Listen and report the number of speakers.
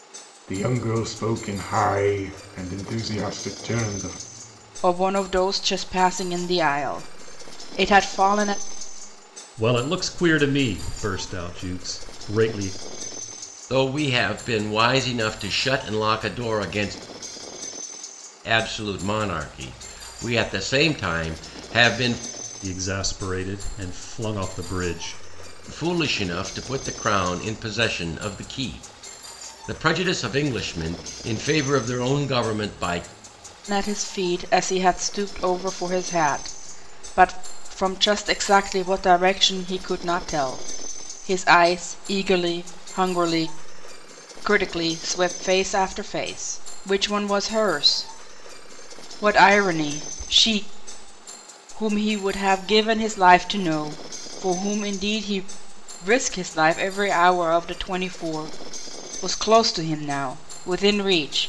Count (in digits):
4